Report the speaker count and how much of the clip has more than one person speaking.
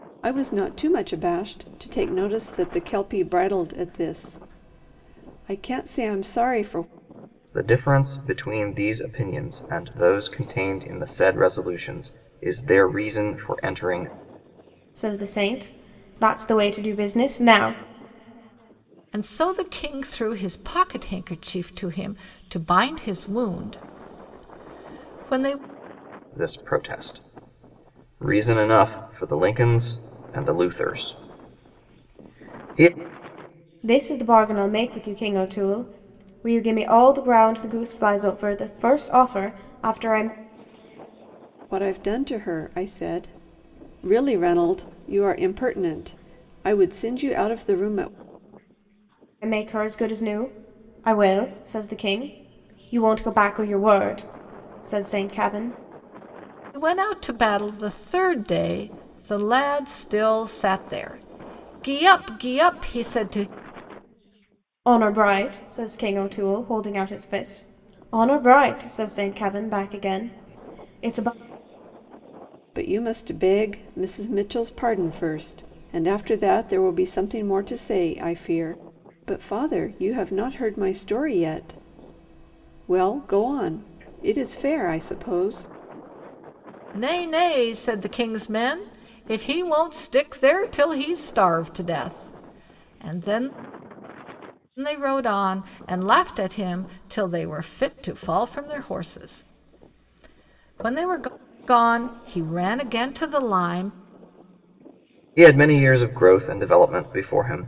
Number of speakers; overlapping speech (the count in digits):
4, no overlap